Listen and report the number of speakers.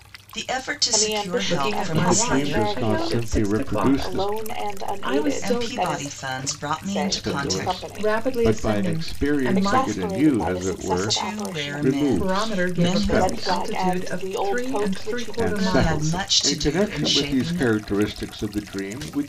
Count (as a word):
four